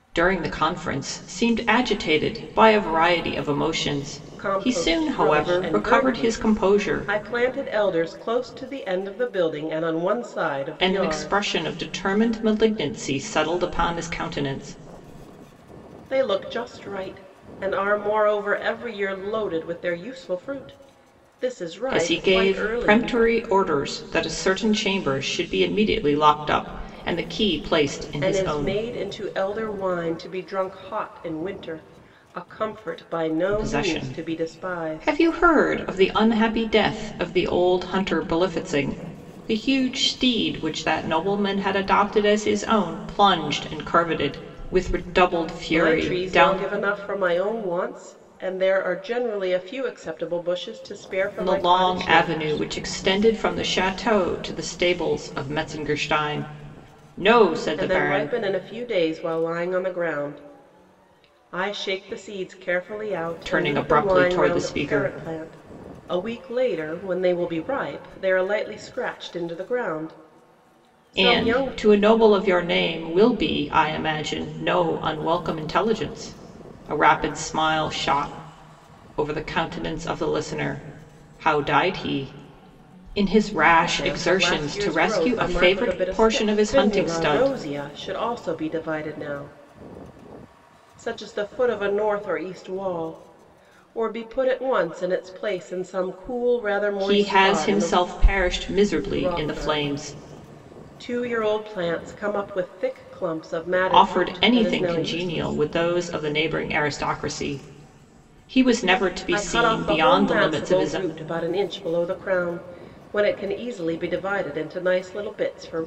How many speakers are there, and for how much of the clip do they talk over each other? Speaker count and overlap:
two, about 18%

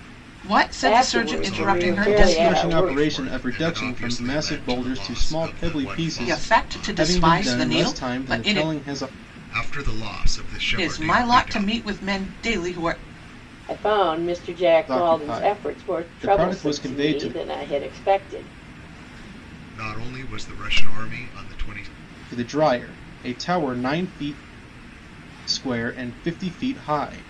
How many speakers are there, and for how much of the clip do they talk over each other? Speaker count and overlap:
four, about 41%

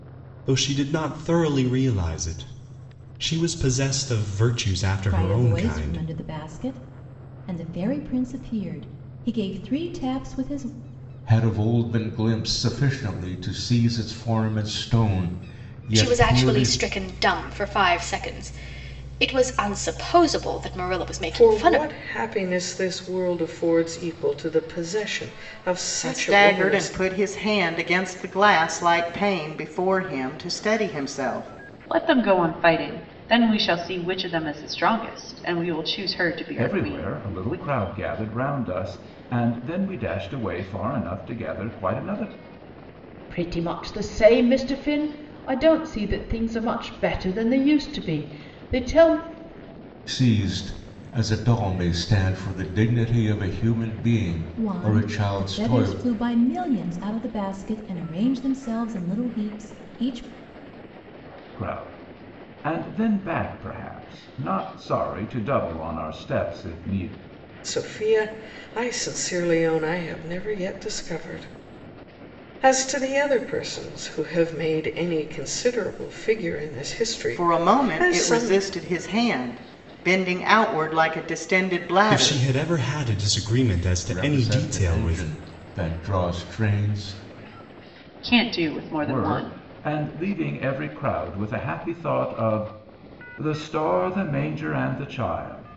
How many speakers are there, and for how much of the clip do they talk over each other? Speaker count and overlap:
nine, about 10%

